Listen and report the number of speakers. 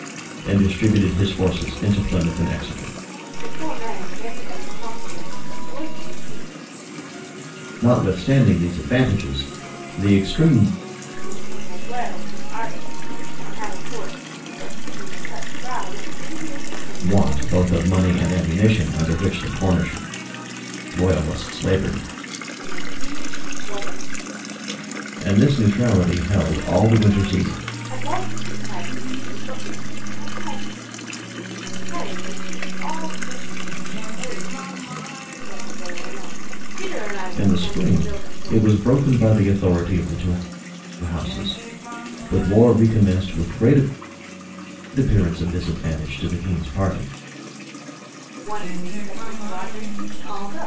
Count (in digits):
2